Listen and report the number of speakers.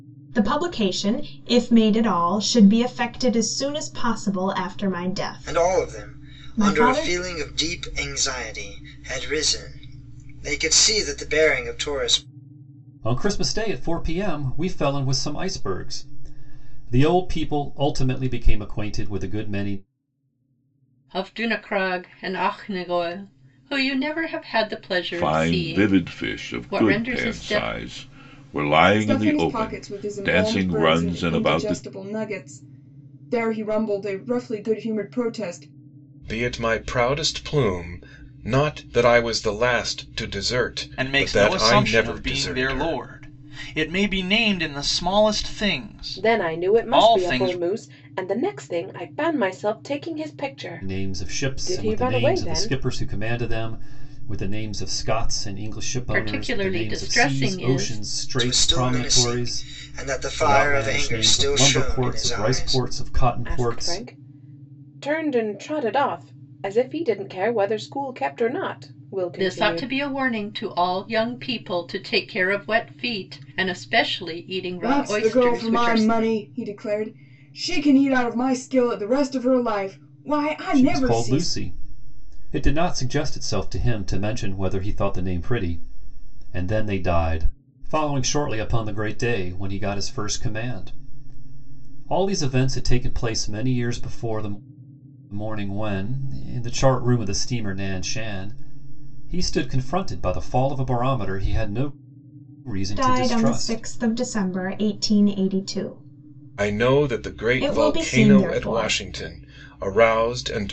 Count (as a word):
nine